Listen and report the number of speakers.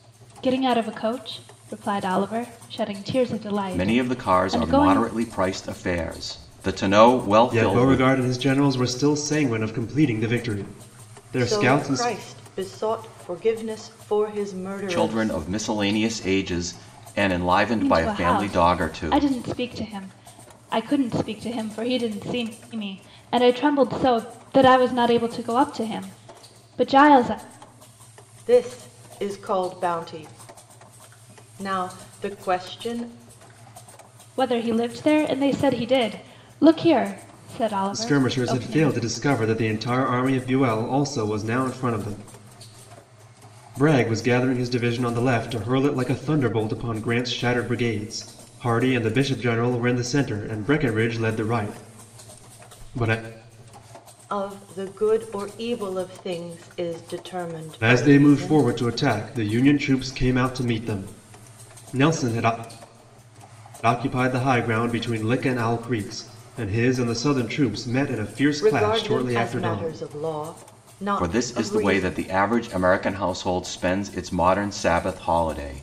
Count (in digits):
4